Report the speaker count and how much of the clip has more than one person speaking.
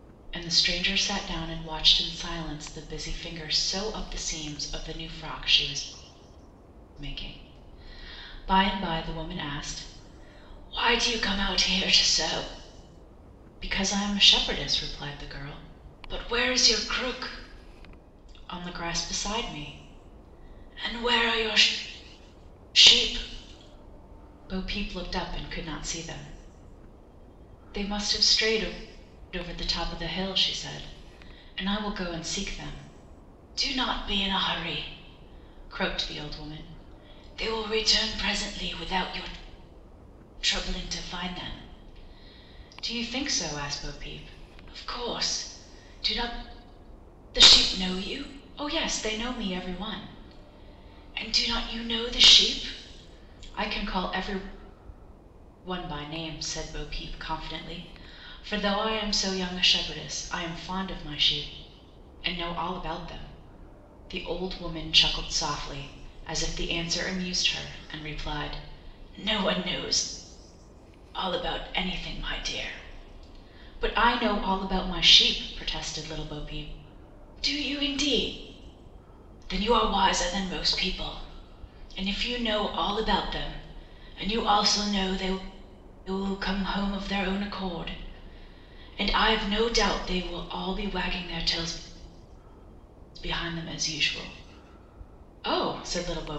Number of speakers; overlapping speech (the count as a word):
one, no overlap